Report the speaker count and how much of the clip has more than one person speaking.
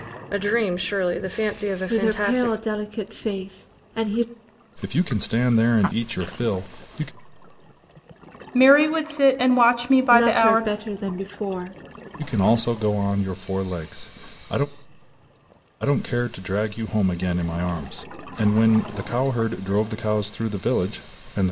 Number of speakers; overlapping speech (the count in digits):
4, about 6%